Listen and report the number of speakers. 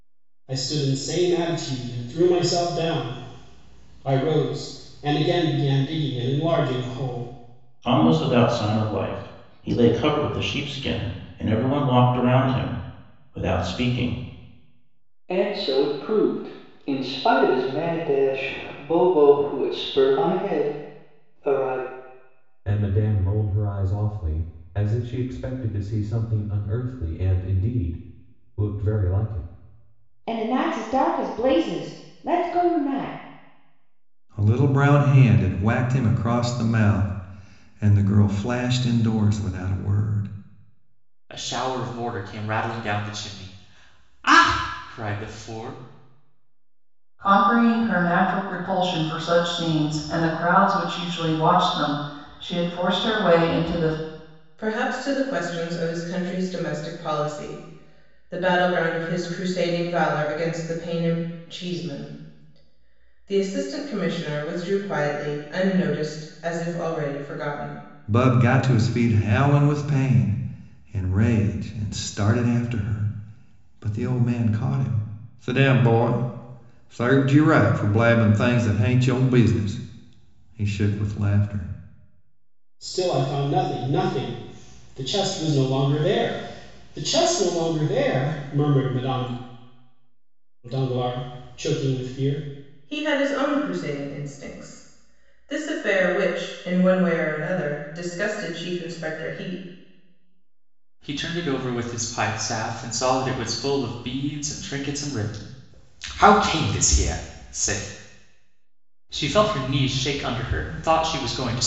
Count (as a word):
nine